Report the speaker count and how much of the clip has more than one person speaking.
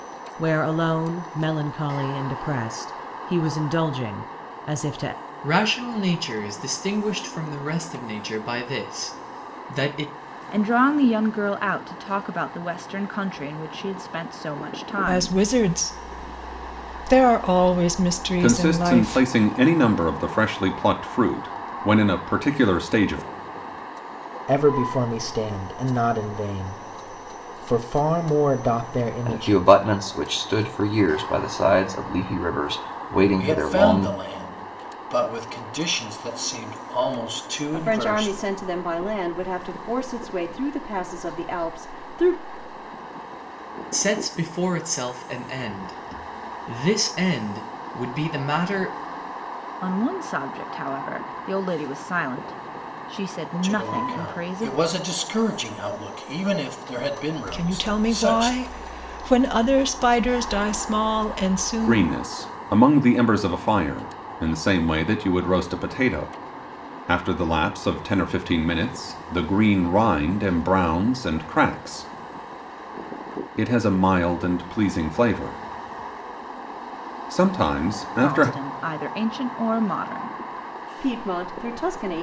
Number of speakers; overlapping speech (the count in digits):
9, about 8%